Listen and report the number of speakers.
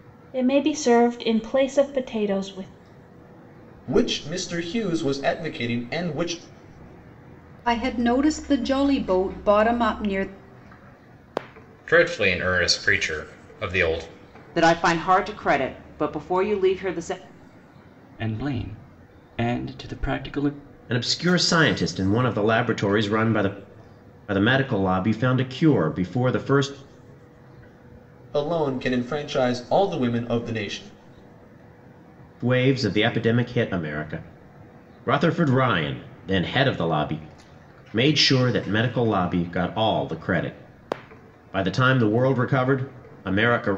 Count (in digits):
7